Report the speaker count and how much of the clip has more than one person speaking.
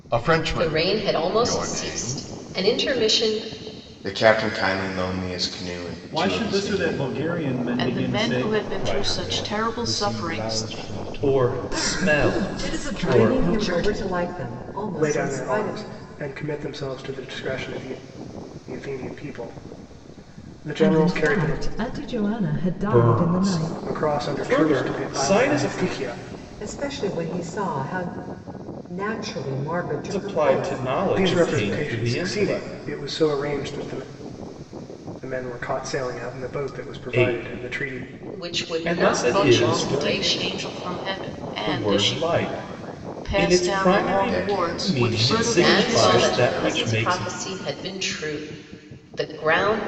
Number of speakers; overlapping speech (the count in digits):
10, about 48%